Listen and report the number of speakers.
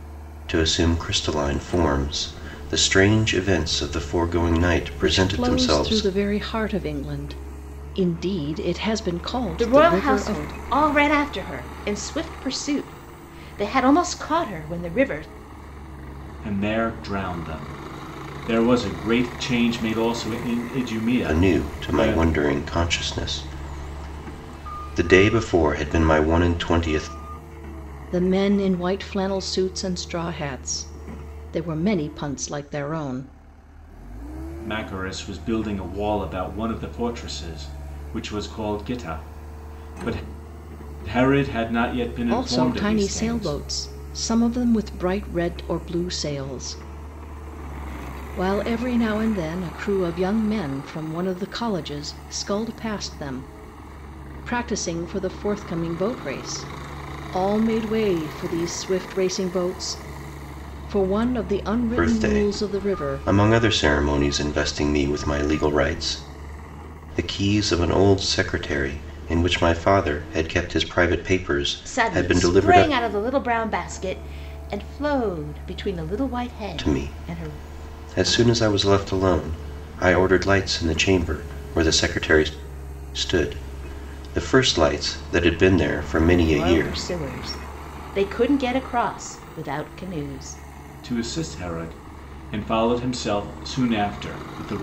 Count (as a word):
four